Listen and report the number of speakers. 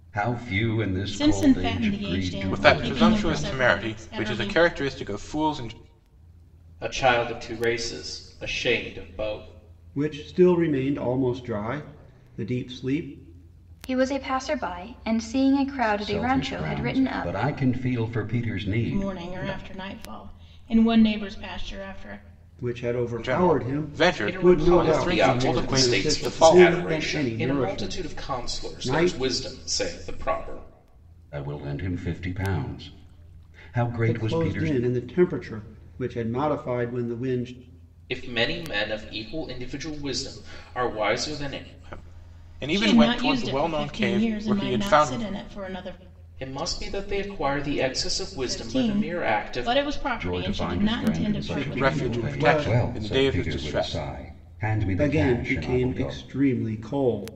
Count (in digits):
6